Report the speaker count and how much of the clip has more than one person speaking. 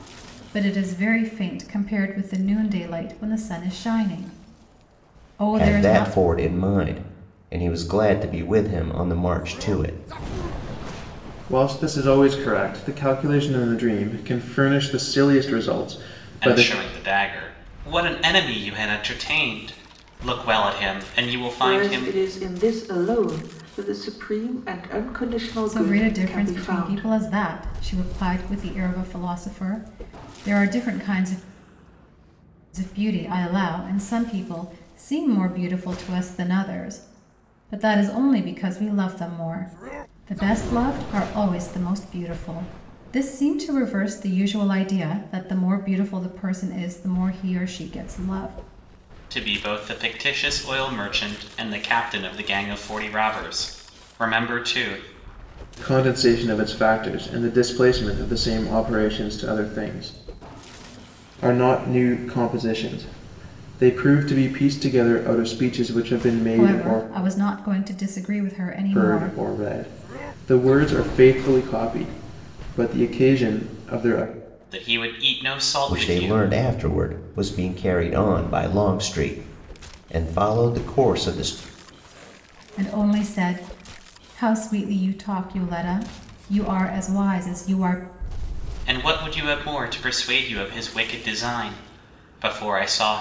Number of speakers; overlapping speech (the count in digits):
5, about 5%